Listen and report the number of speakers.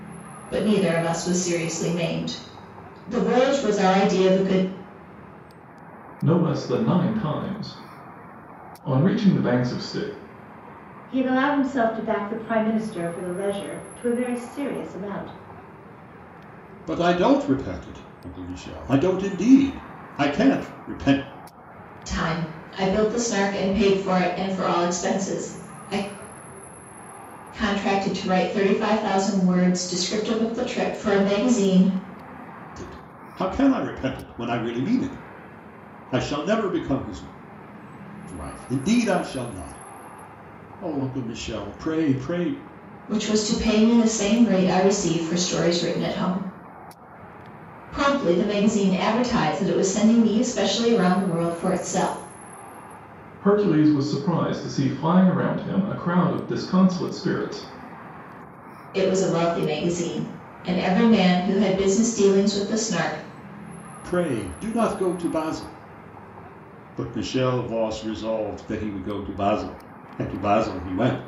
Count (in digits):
4